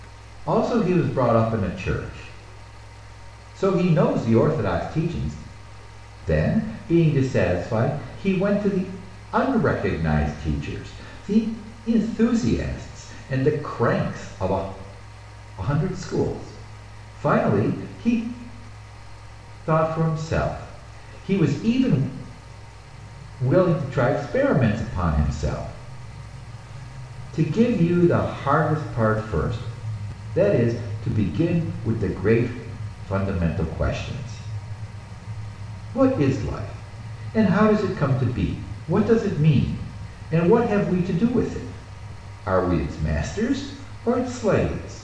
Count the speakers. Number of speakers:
1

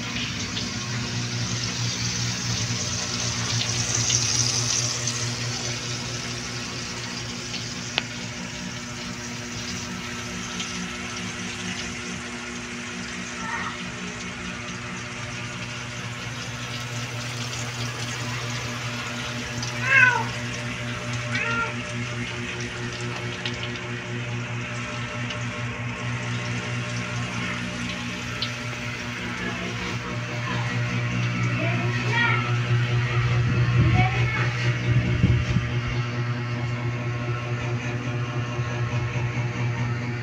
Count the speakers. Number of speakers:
0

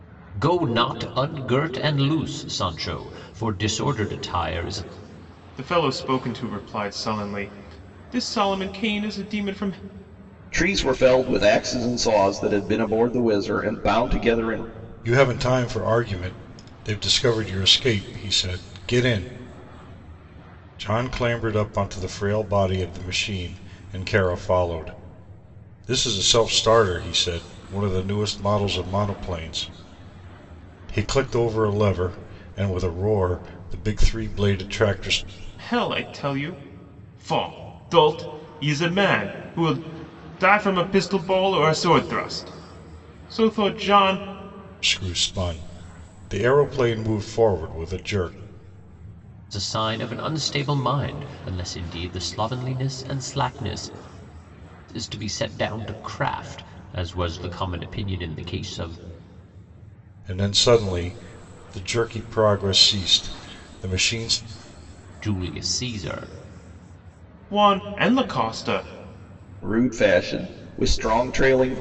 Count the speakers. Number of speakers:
4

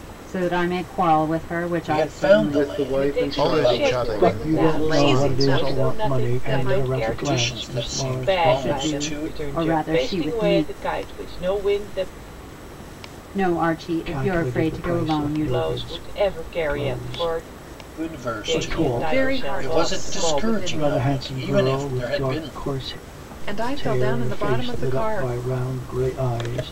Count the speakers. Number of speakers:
7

